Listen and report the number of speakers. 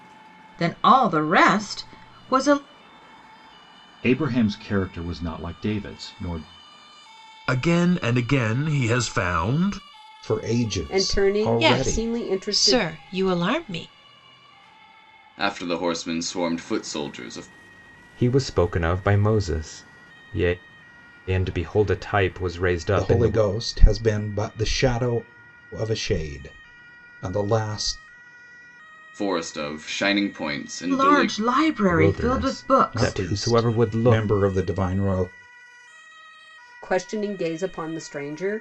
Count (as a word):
eight